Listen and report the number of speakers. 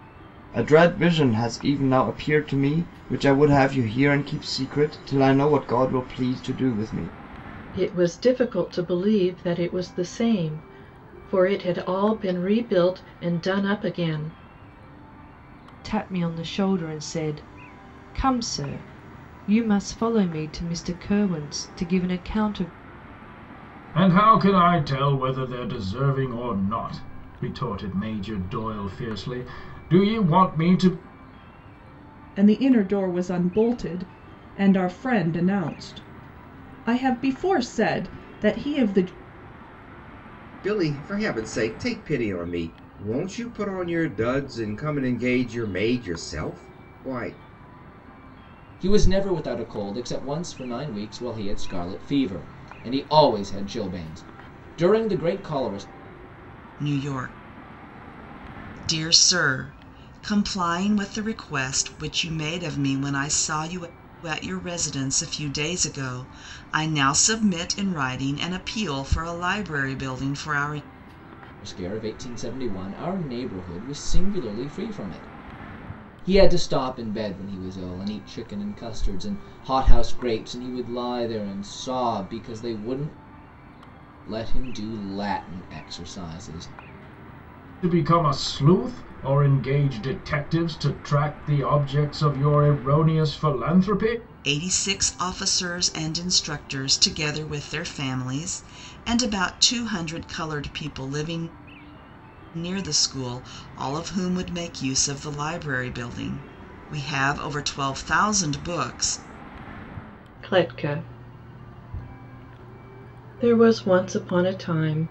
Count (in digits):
8